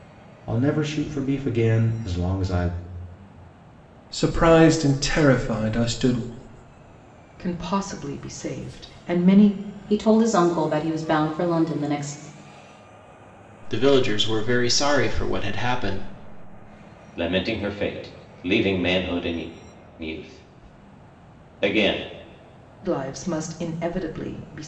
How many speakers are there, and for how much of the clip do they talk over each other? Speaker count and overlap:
6, no overlap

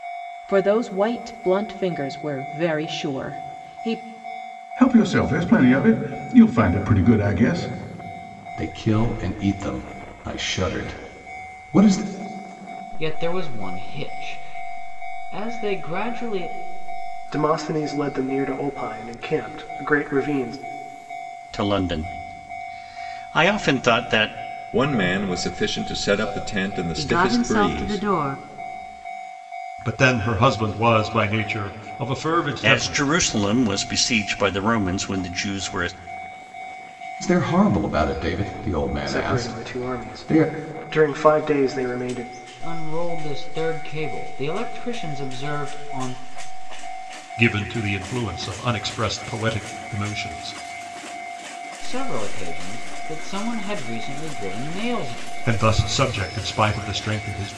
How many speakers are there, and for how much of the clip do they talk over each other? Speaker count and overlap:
9, about 6%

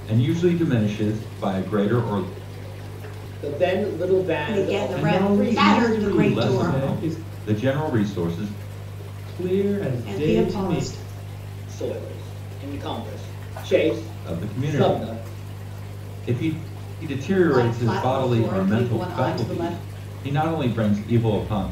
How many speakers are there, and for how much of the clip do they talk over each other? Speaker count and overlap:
4, about 33%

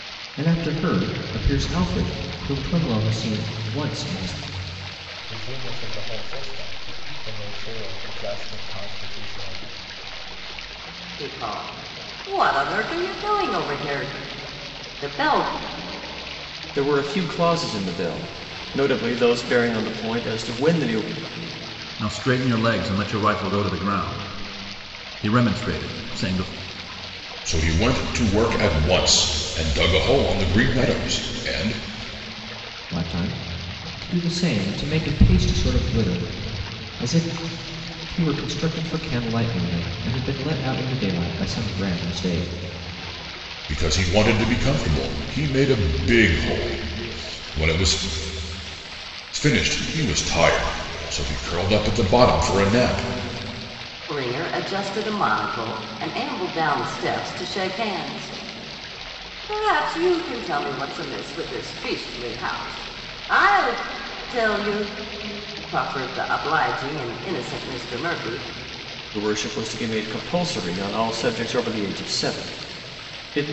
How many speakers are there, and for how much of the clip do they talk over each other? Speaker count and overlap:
6, no overlap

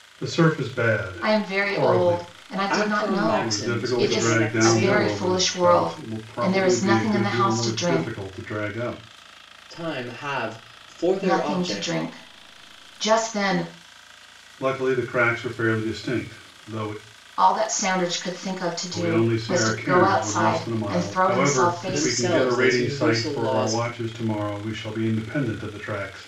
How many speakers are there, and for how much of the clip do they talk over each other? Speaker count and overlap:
3, about 46%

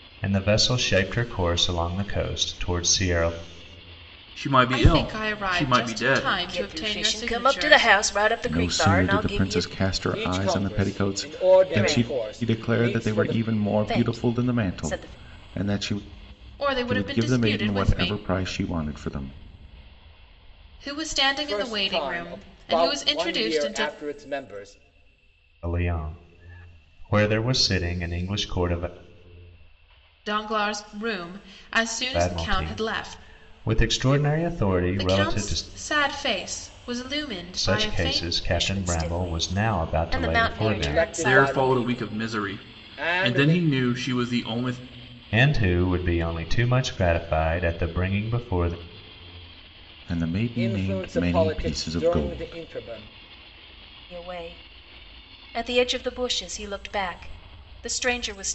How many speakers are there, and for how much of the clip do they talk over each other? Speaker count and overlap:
6, about 40%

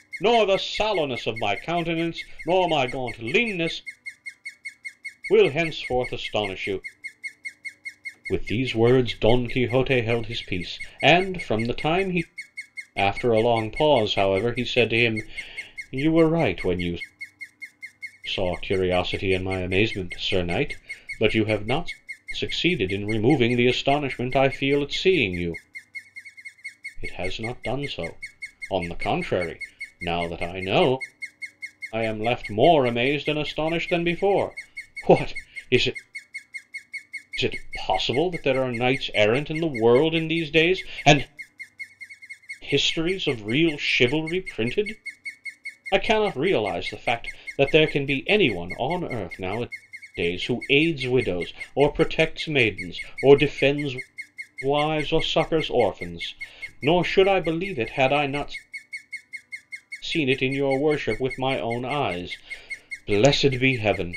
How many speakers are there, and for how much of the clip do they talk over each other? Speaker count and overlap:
1, no overlap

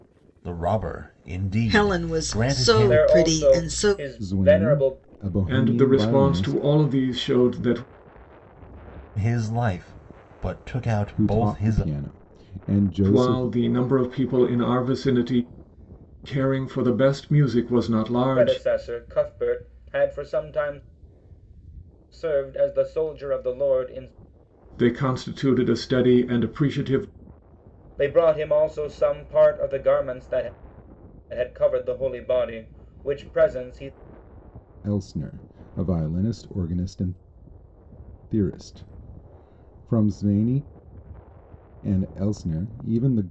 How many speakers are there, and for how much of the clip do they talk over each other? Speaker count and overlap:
5, about 14%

